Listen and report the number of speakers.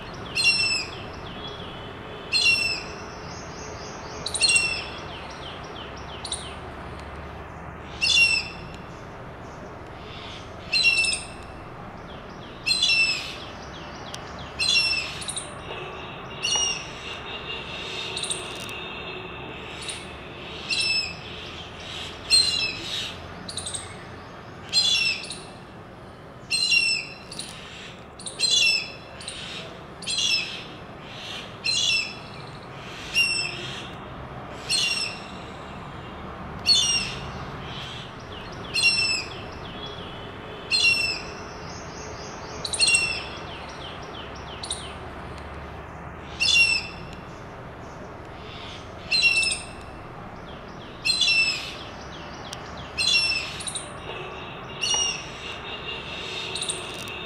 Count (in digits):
0